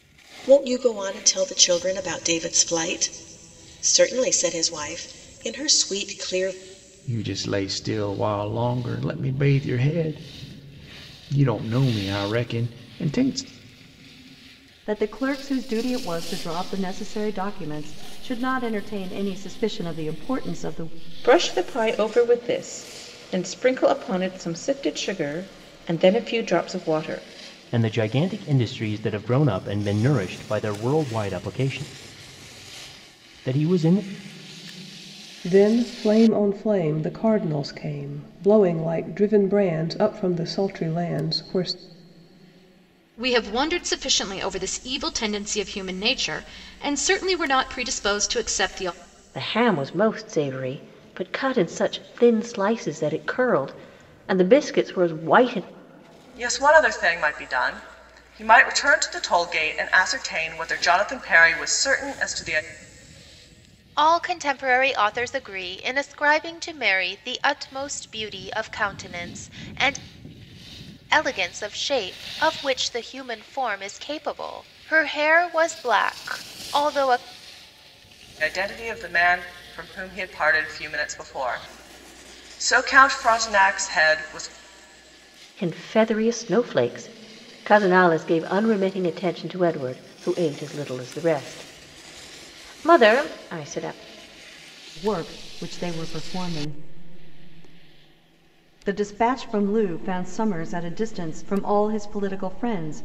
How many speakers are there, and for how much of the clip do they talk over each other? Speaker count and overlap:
ten, no overlap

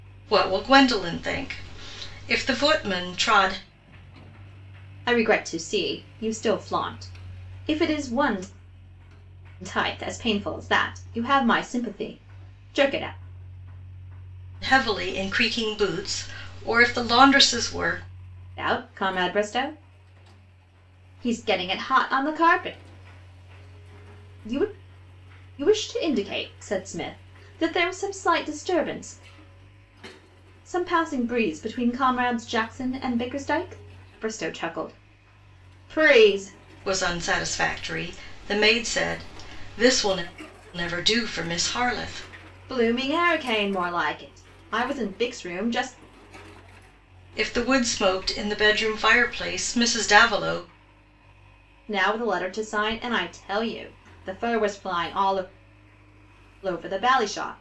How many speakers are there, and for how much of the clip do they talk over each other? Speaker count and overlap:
two, no overlap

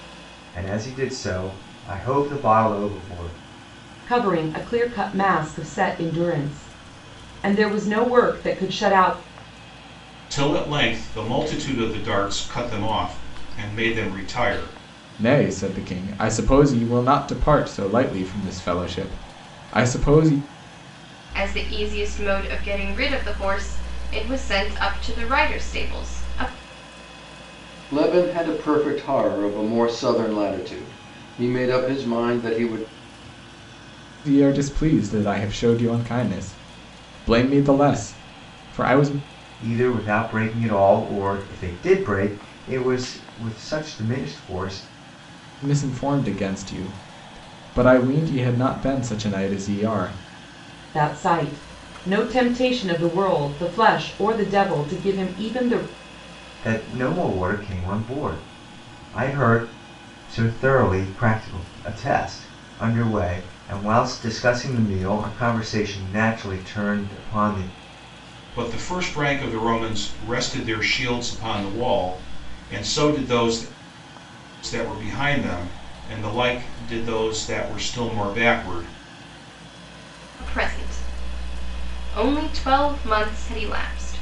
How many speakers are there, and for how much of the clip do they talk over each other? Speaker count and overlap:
six, no overlap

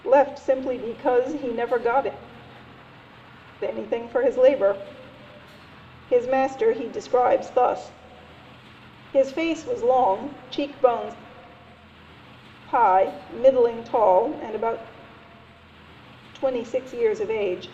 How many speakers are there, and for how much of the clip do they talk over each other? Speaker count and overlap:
one, no overlap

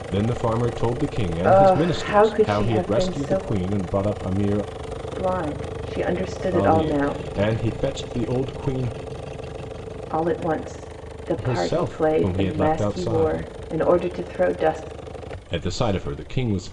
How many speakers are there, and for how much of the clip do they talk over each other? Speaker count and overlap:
two, about 29%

